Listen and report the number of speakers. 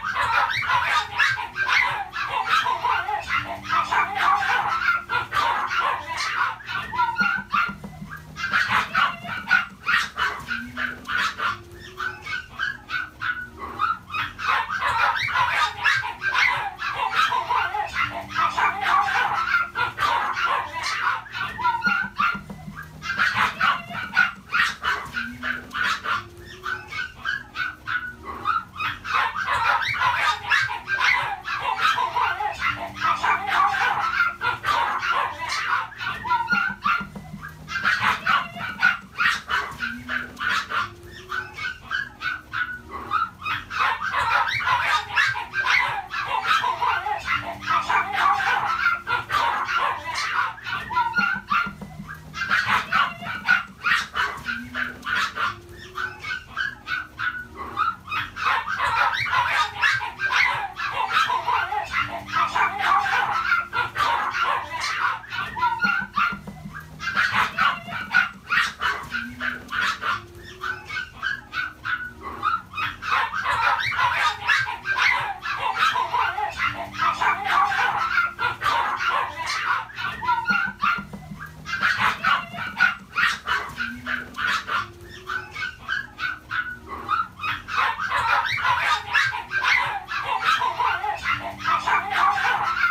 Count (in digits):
0